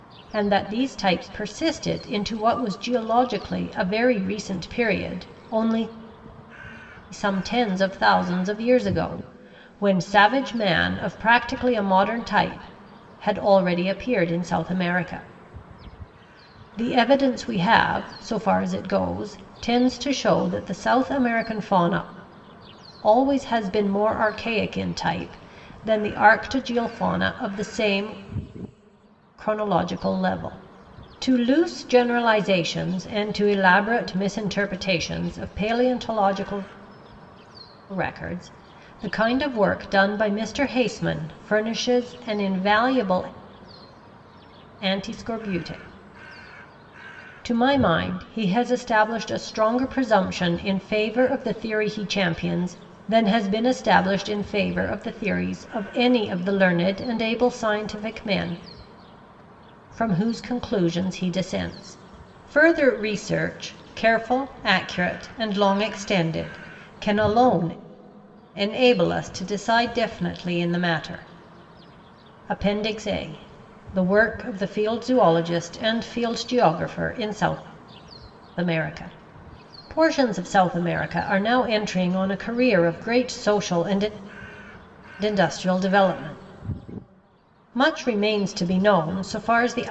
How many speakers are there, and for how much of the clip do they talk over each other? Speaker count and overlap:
1, no overlap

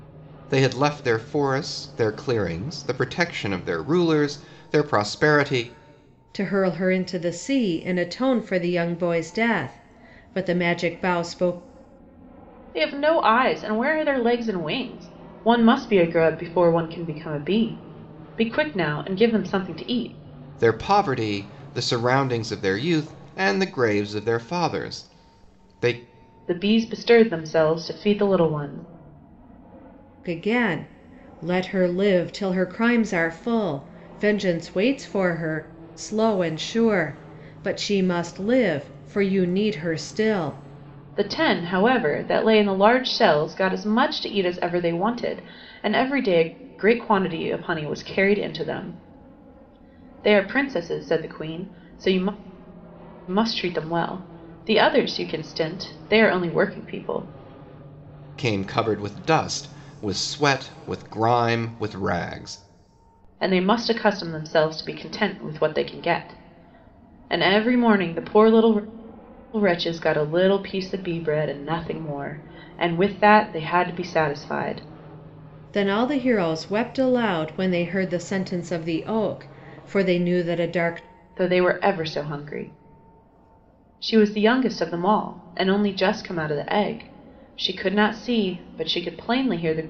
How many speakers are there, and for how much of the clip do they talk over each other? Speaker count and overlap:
3, no overlap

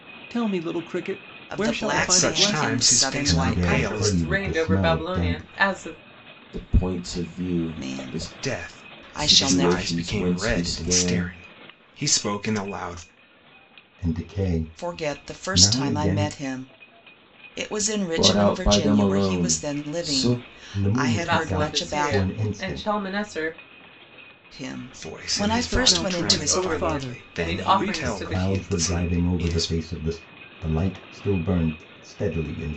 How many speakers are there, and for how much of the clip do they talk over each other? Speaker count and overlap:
6, about 56%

